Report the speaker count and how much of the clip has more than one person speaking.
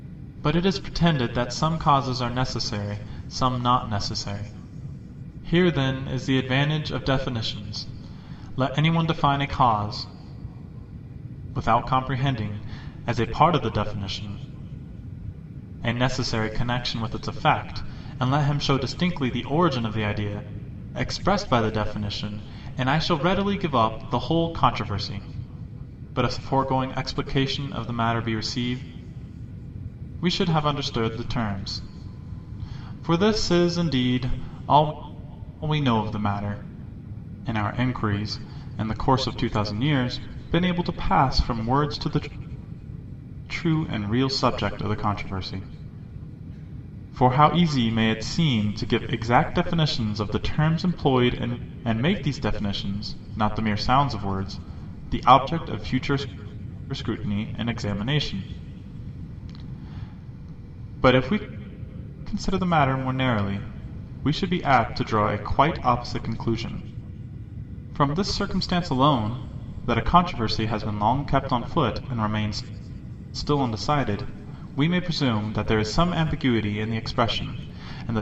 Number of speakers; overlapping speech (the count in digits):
1, no overlap